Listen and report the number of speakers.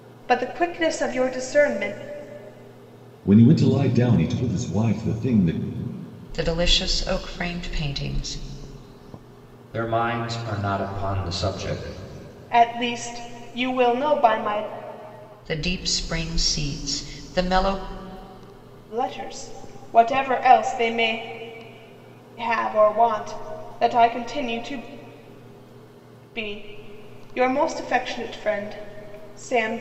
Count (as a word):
four